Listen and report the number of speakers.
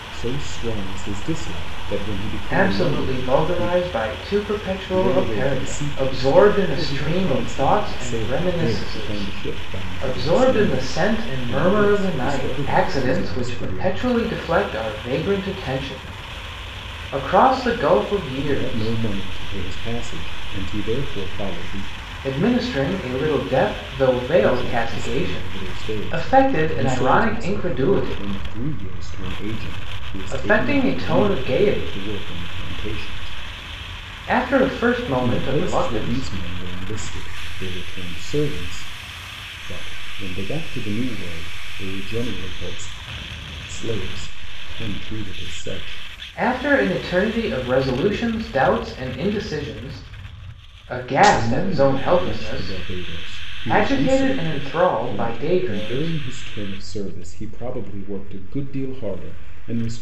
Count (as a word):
two